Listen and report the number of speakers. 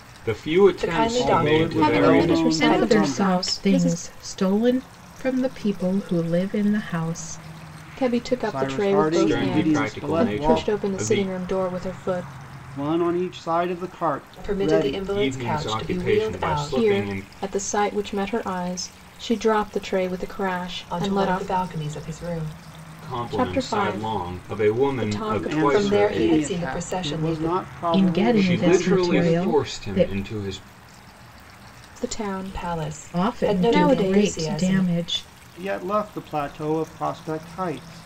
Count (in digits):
5